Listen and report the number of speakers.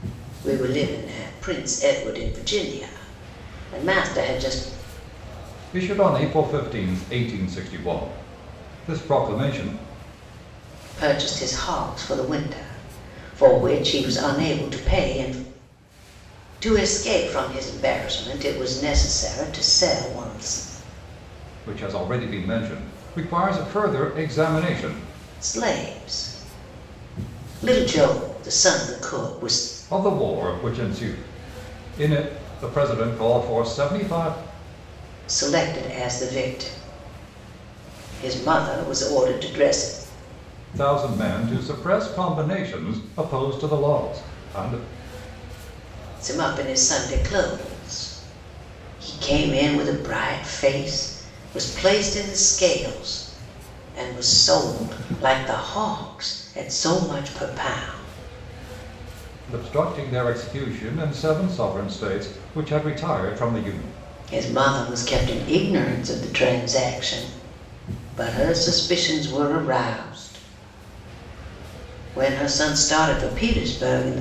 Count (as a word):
two